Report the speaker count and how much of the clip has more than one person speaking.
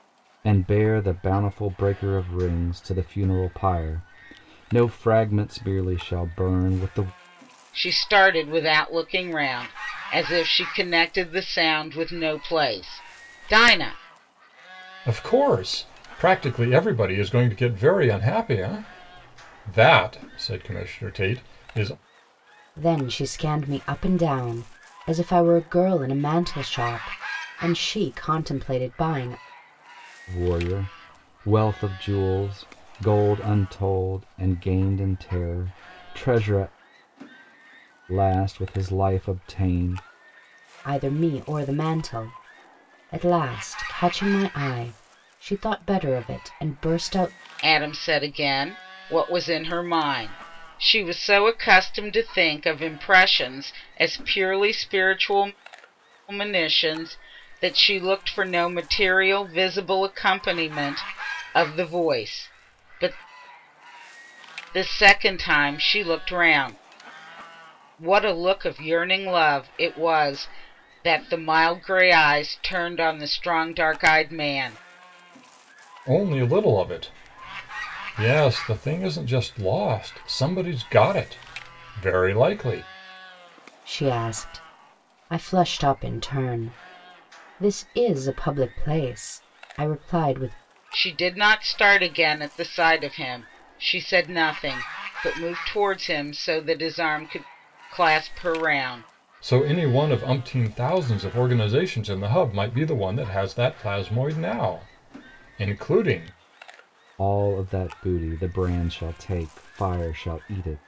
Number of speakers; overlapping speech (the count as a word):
four, no overlap